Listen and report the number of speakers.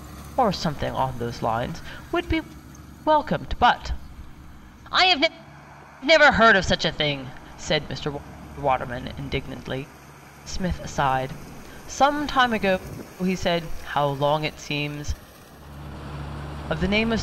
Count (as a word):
one